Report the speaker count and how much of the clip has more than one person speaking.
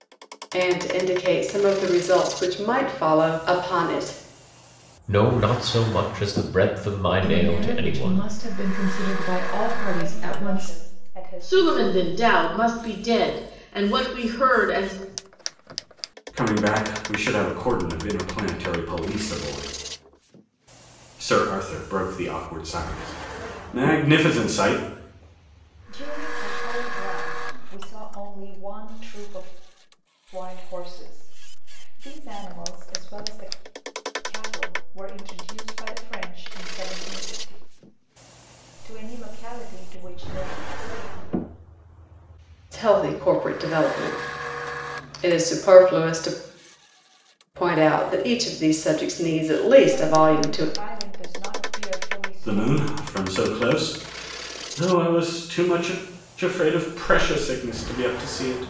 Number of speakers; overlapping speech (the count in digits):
6, about 8%